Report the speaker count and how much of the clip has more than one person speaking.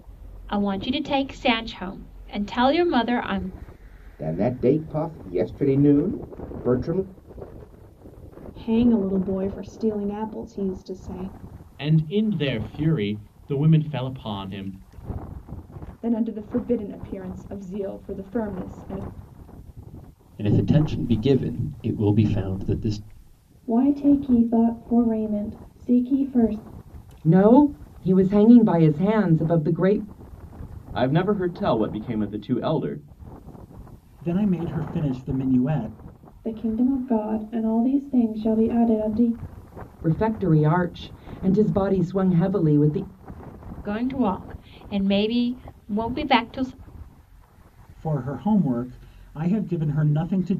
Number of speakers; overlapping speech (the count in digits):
10, no overlap